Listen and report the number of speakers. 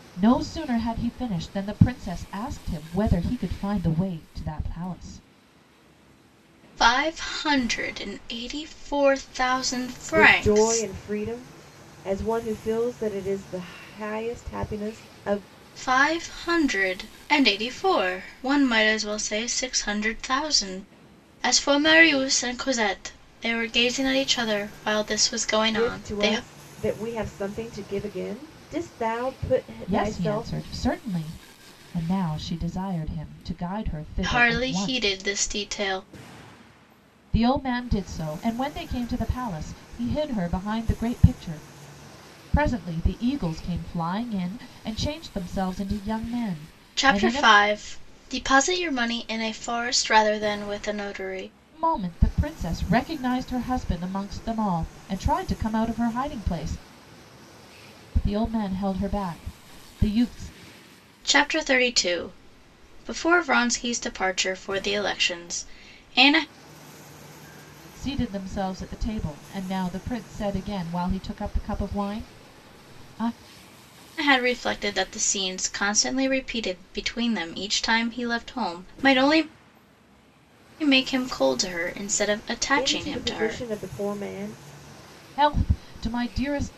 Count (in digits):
3